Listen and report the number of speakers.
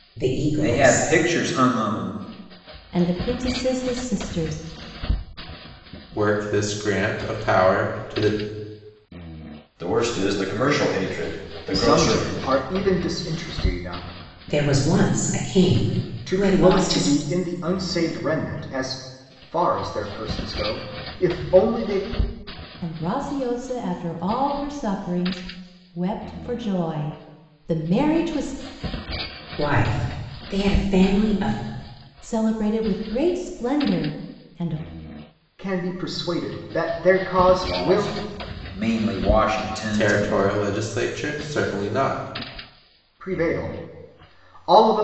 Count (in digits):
6